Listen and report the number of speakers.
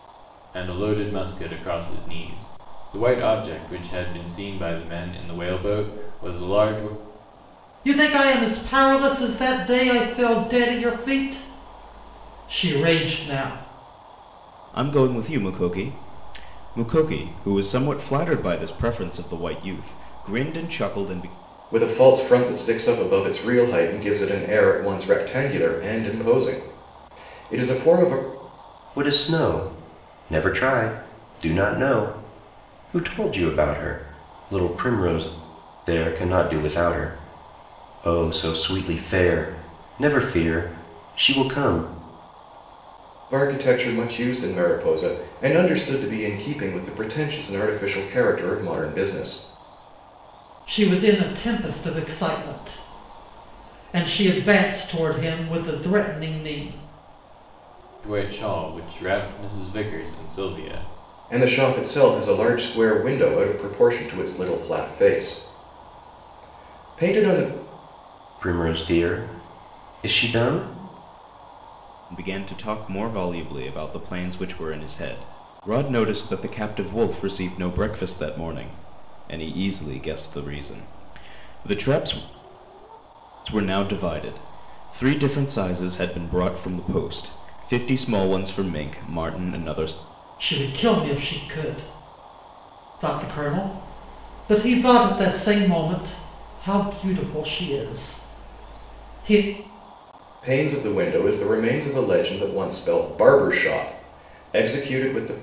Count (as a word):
five